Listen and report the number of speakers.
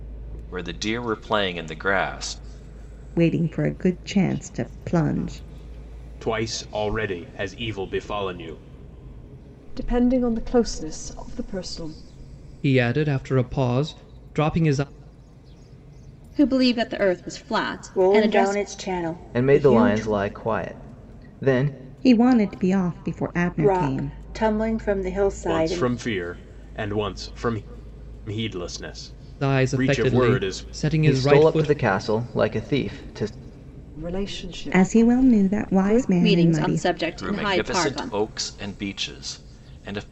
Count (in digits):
8